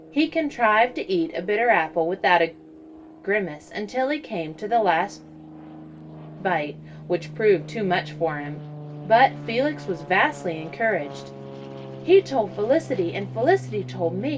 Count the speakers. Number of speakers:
1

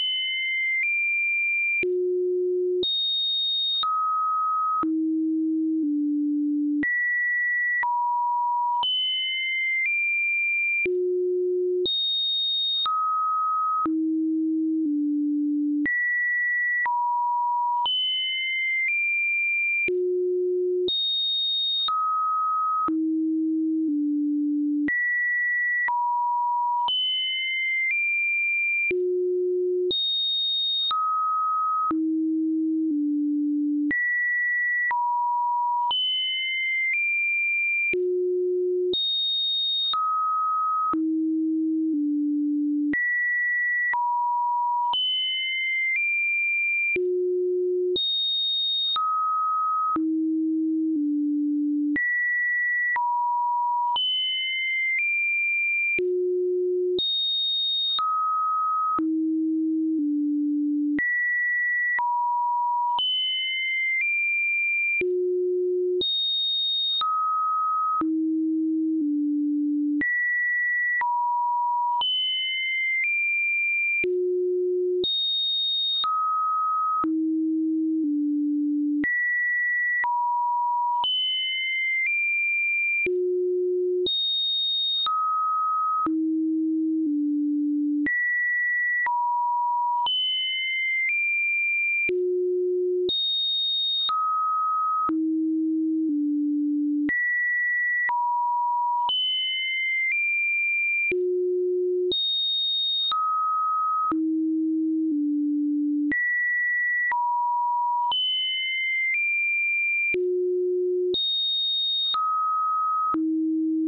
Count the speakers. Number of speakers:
0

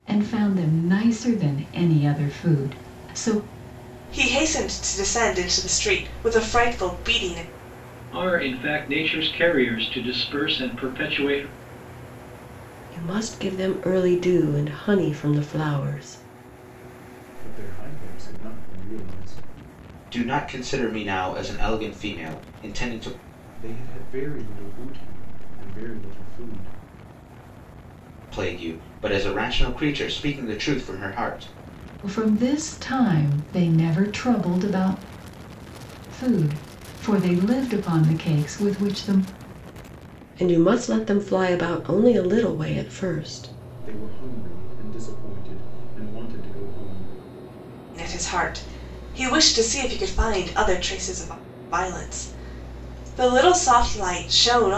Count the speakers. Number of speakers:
6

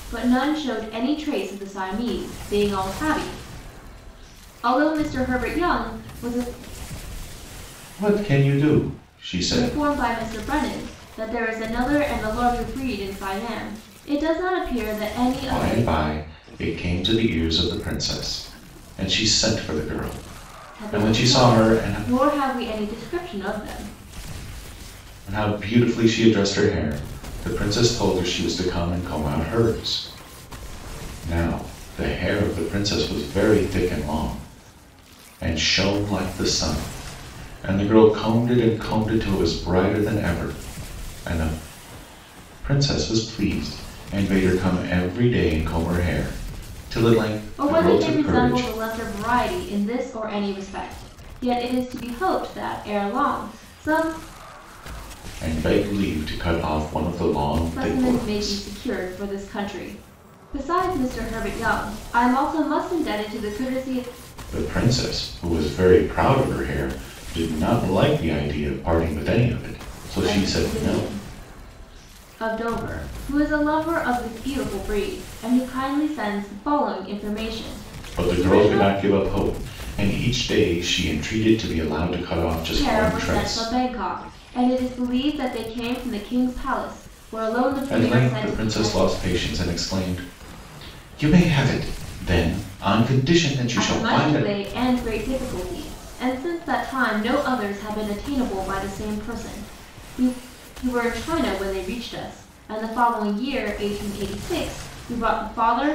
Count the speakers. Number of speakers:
2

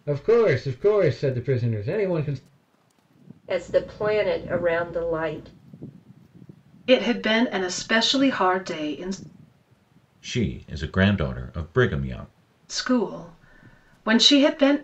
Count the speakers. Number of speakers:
4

